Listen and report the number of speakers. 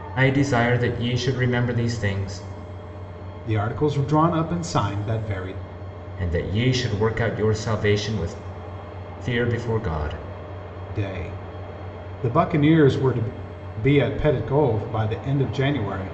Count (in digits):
2